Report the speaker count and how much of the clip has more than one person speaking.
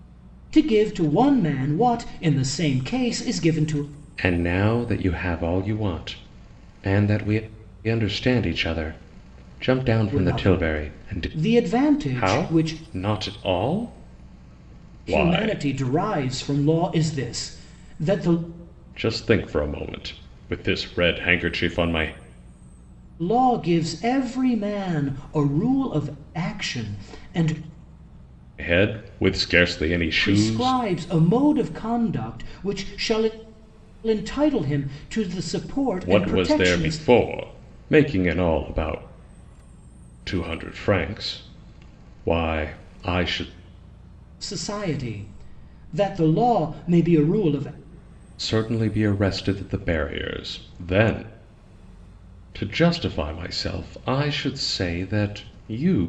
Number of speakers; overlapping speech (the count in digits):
2, about 7%